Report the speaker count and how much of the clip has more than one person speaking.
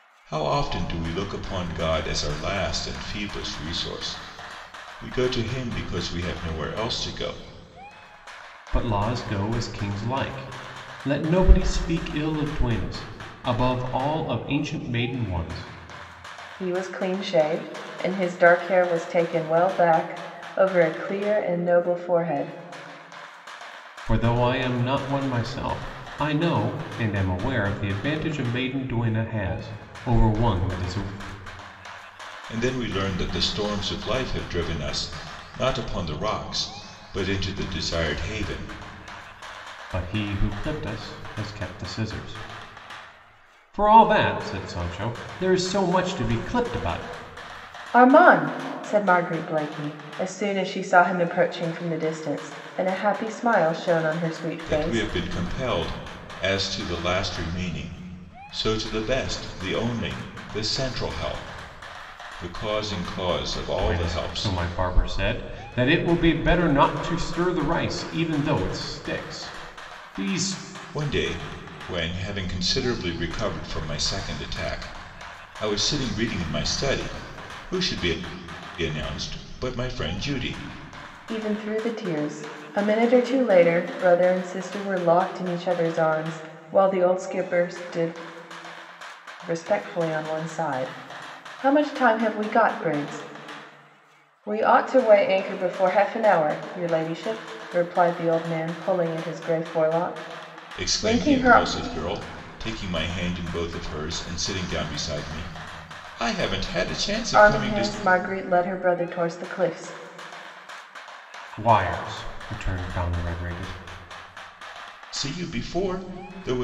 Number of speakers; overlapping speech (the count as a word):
three, about 2%